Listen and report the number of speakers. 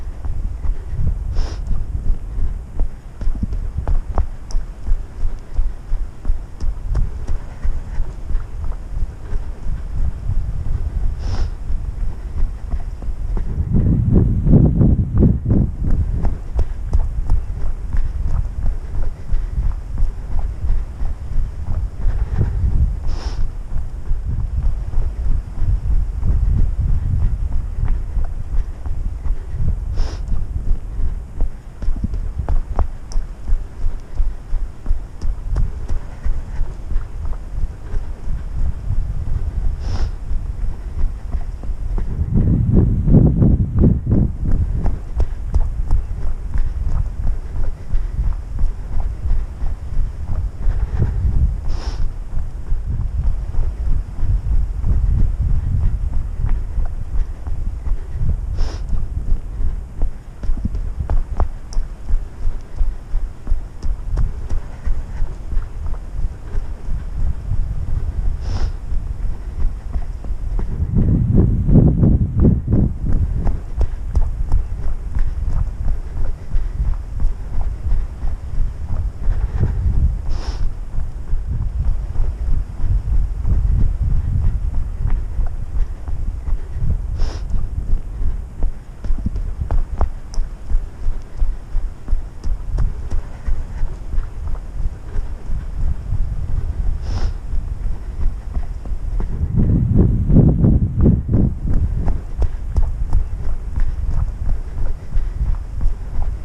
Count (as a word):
zero